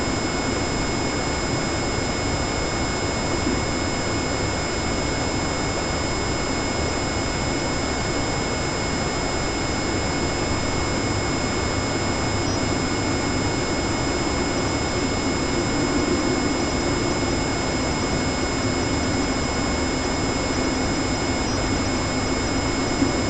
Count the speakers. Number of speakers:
0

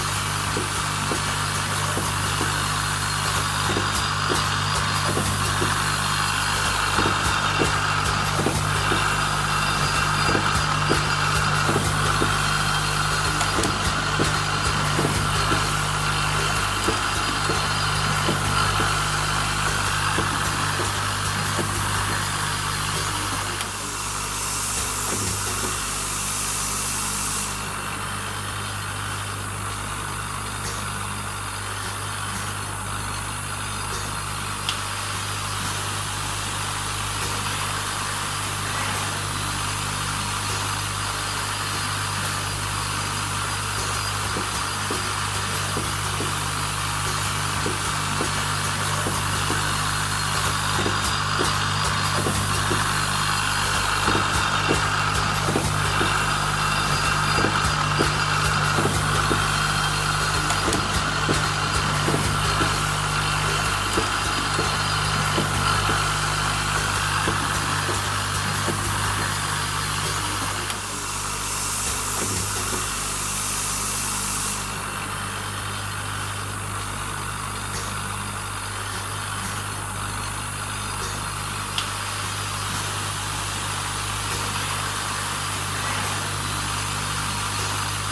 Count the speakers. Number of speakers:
0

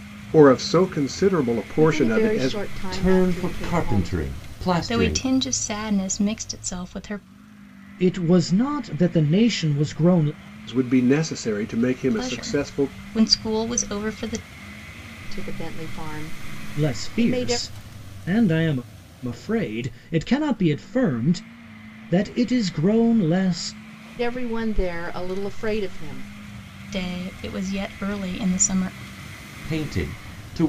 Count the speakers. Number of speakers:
5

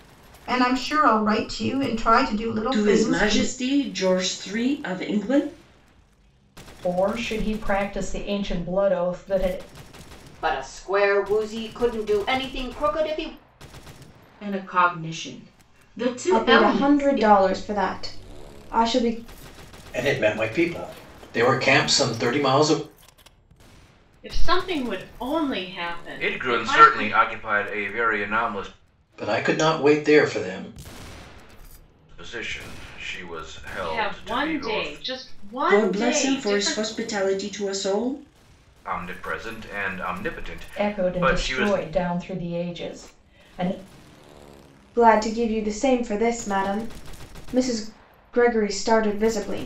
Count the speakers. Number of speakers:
9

